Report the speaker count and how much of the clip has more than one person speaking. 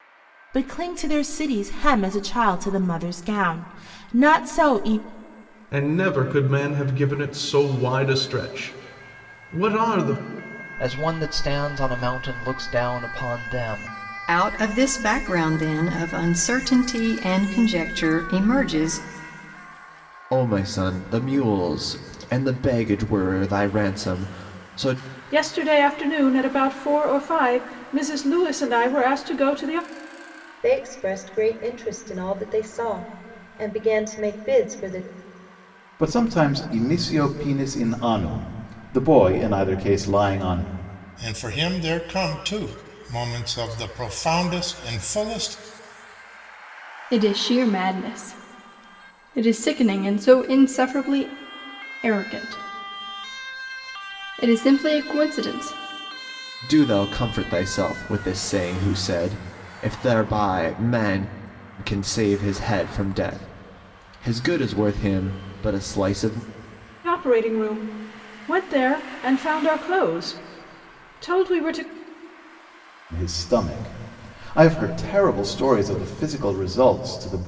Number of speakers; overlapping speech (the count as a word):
ten, no overlap